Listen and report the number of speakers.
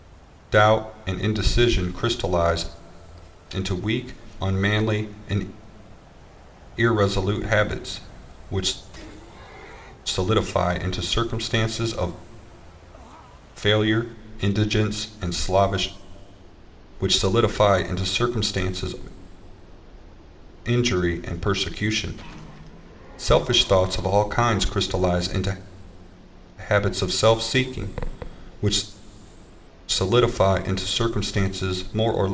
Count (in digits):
1